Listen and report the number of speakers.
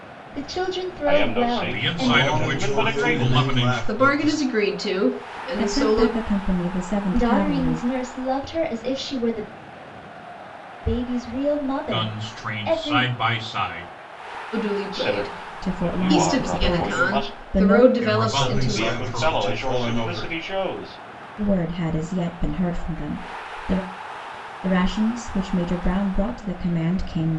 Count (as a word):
six